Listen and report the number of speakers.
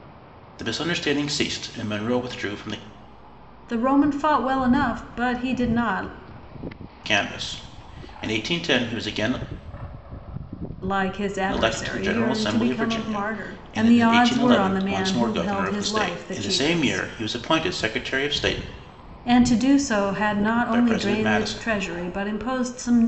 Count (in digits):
2